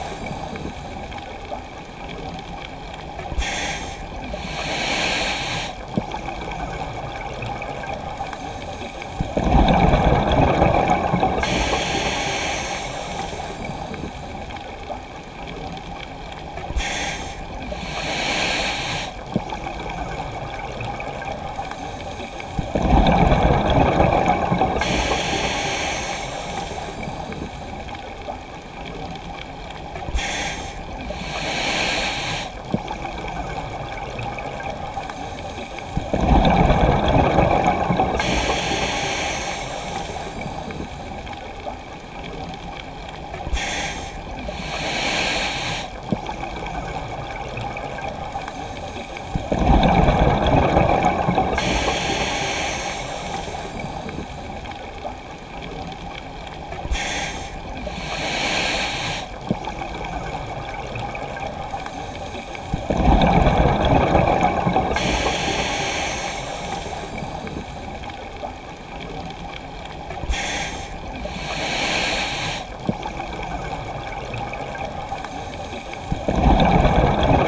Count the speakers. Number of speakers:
zero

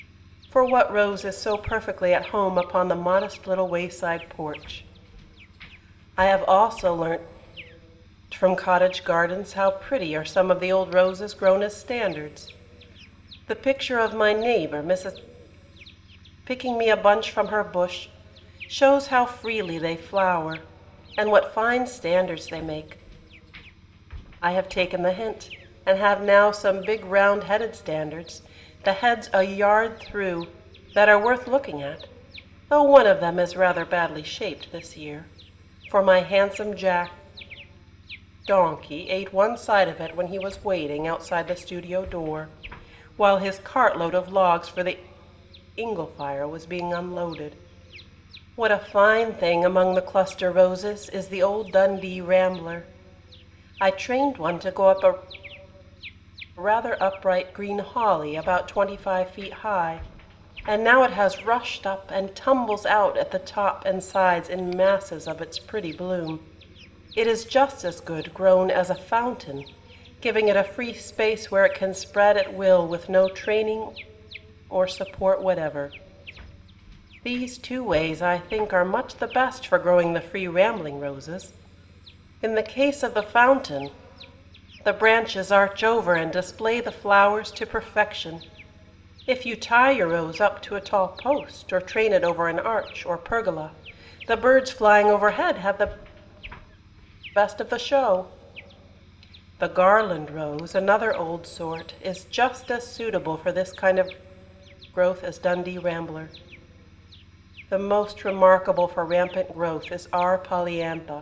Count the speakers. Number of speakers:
one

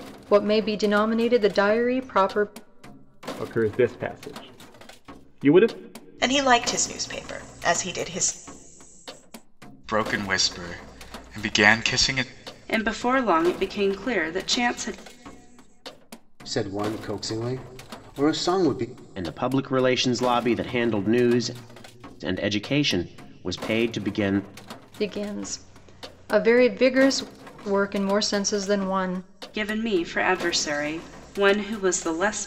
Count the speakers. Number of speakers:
seven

